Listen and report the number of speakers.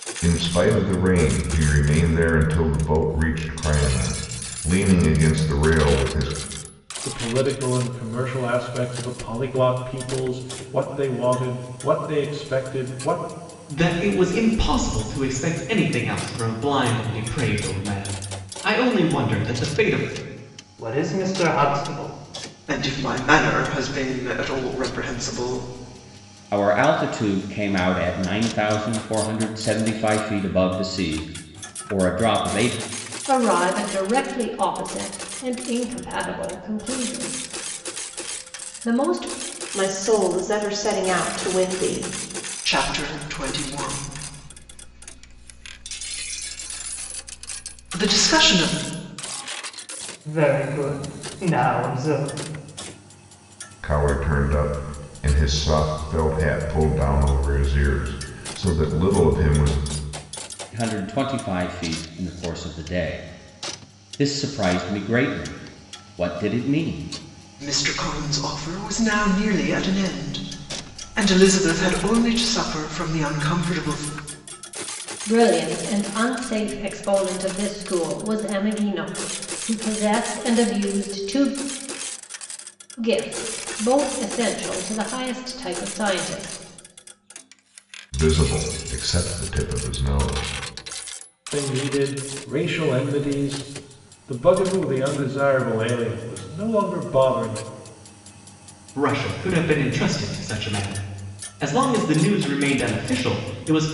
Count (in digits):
8